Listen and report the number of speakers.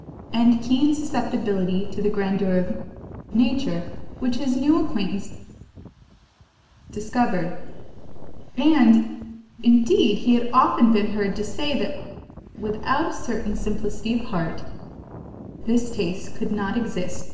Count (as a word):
one